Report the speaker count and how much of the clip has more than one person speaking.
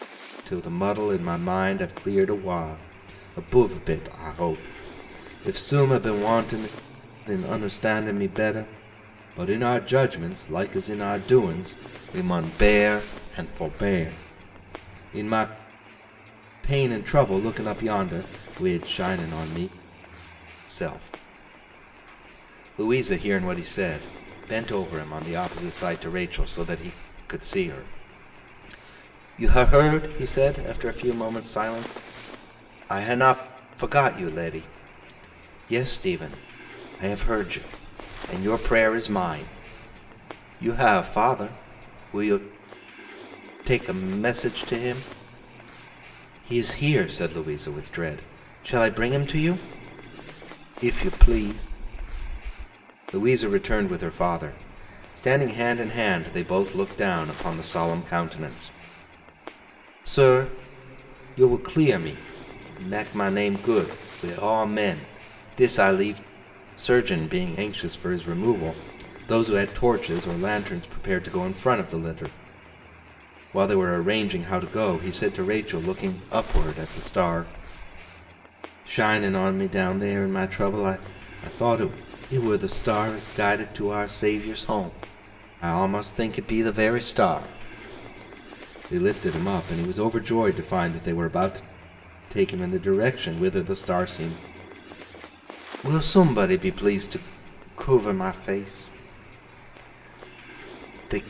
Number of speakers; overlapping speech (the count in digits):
1, no overlap